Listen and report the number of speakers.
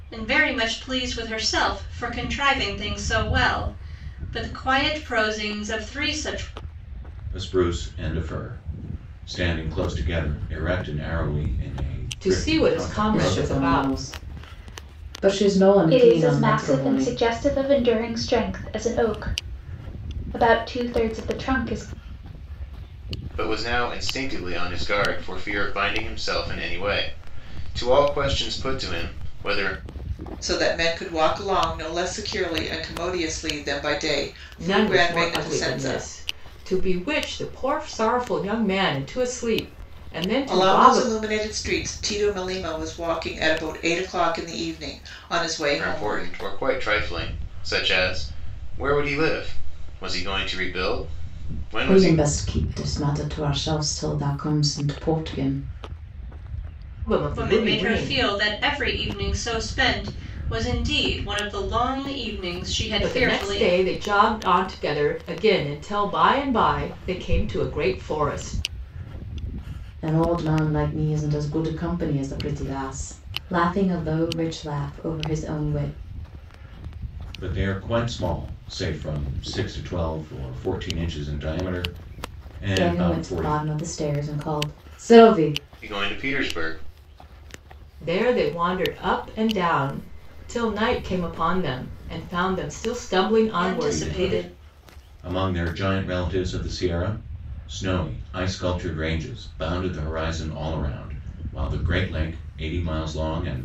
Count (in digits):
7